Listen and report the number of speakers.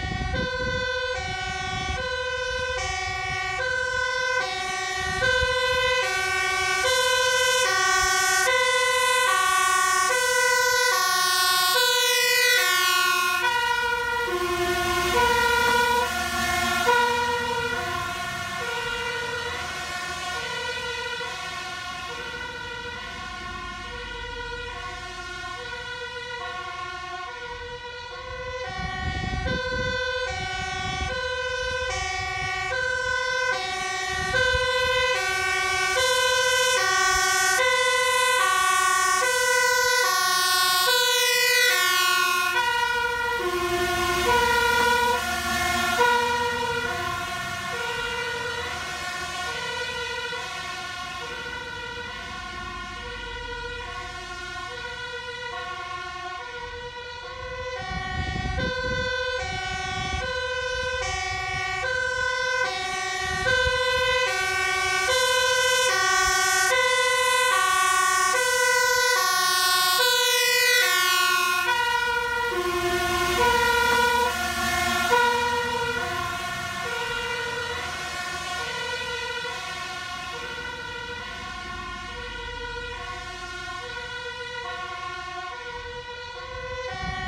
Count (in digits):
0